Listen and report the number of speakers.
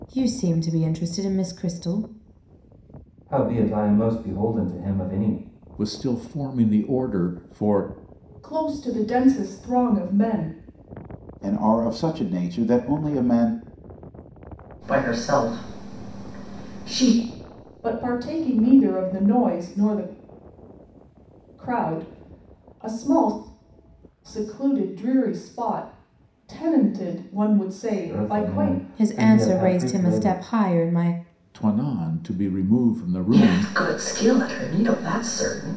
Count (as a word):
six